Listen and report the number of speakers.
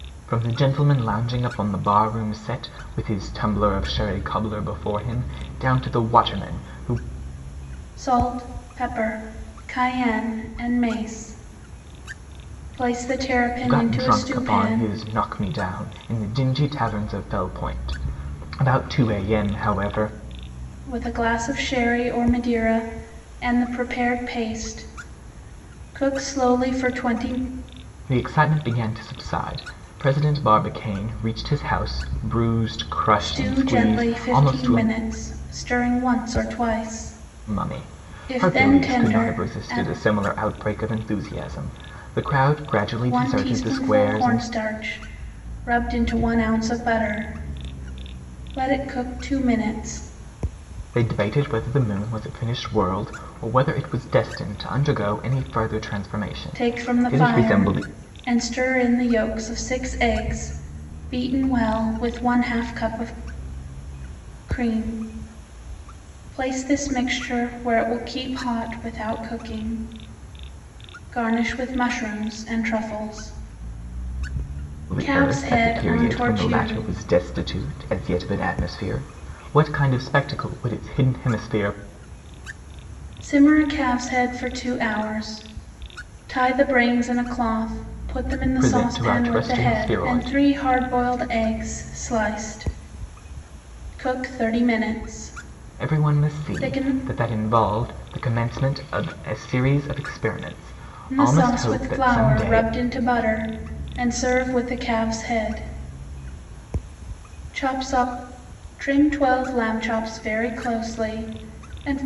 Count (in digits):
2